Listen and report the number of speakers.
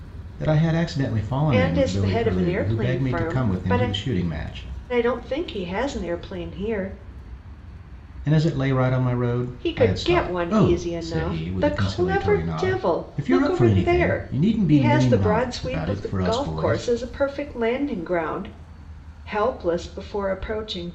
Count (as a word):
two